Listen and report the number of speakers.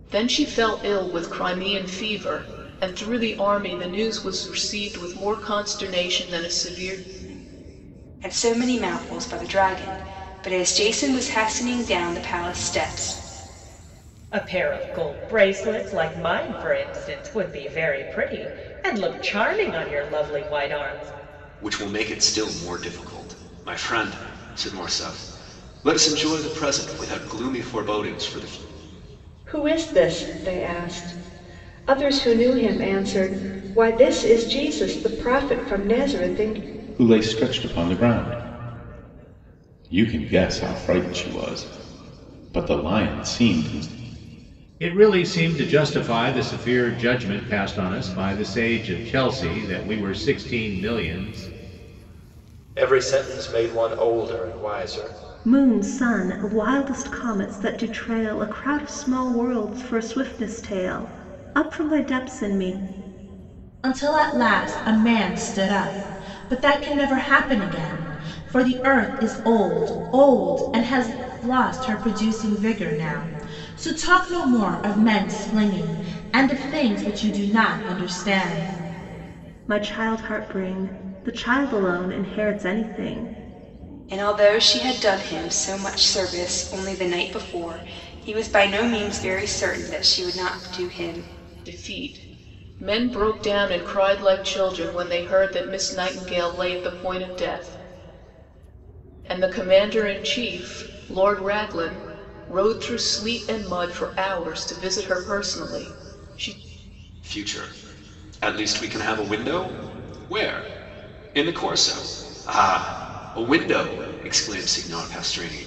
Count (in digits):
10